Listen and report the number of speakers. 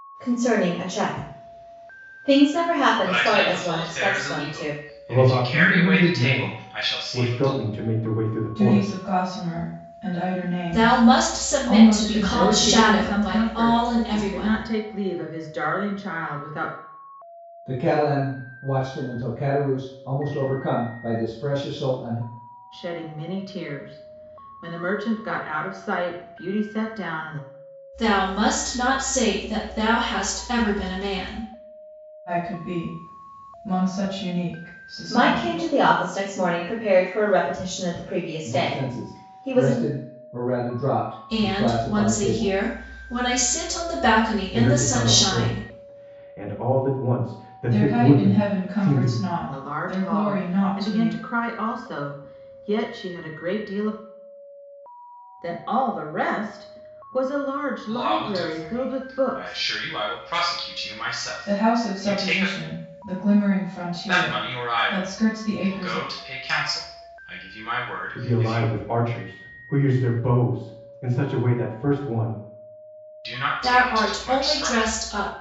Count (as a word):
seven